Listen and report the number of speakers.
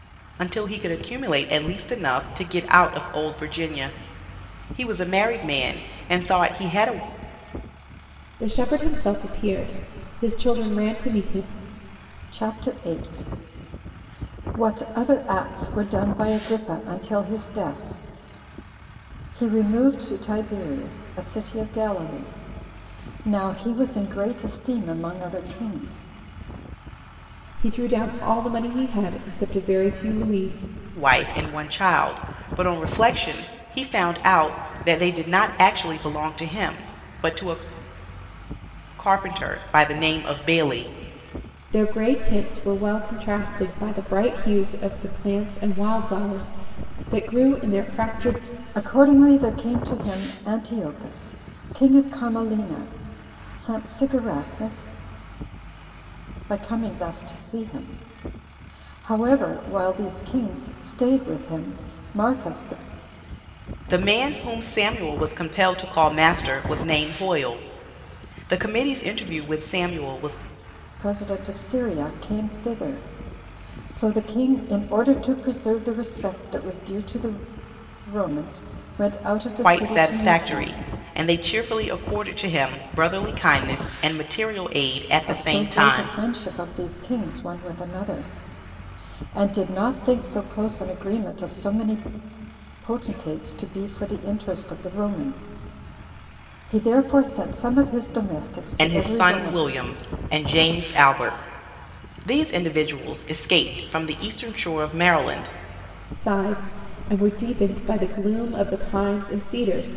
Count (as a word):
three